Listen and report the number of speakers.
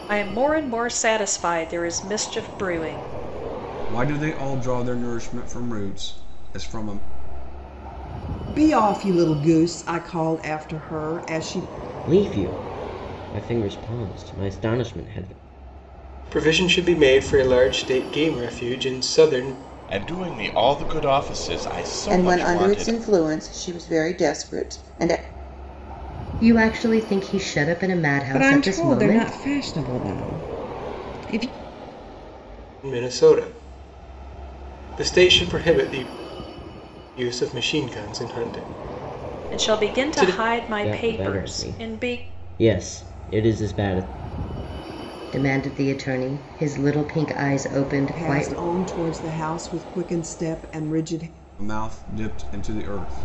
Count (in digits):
9